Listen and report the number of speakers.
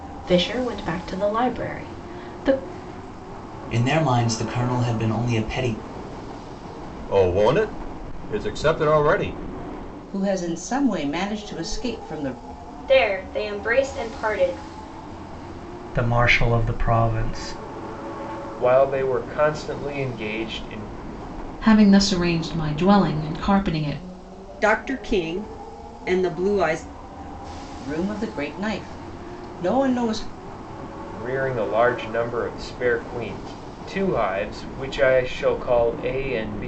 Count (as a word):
nine